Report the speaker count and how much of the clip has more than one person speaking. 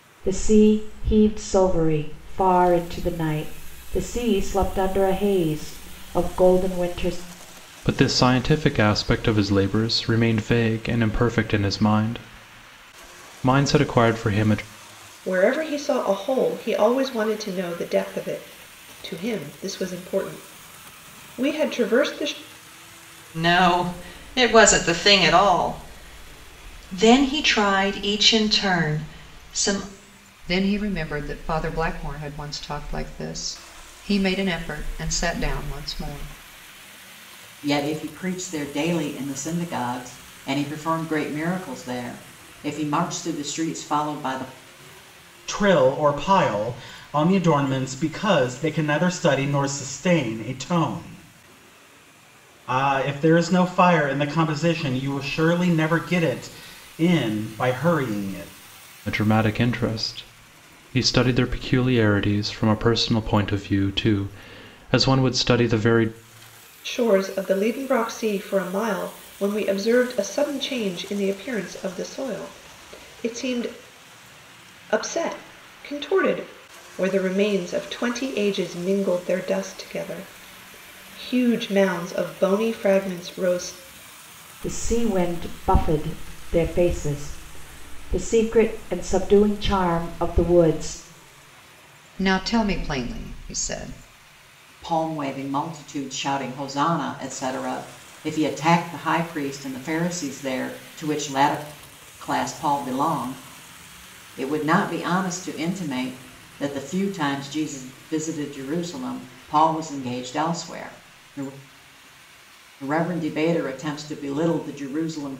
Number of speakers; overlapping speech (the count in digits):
7, no overlap